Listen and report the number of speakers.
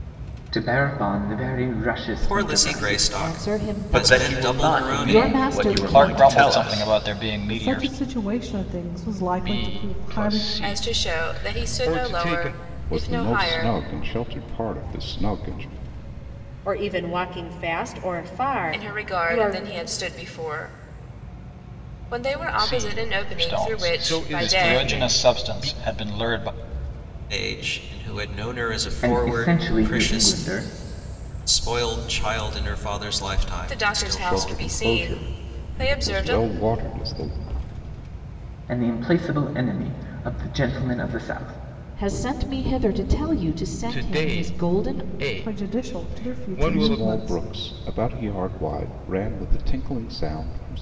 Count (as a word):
ten